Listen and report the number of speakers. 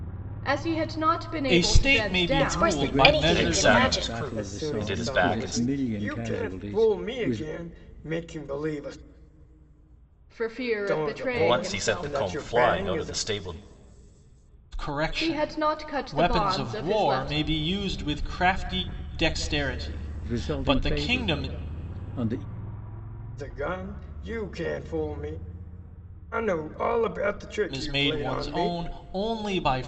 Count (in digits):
6